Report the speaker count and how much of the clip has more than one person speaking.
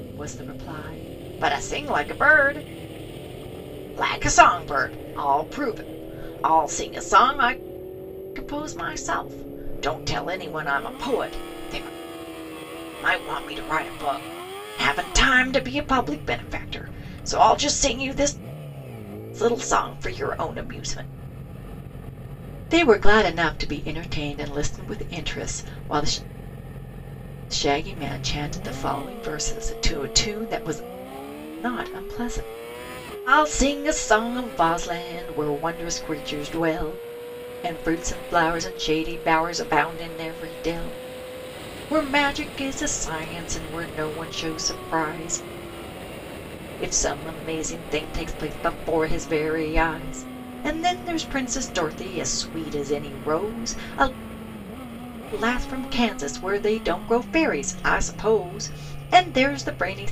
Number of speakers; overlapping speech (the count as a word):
one, no overlap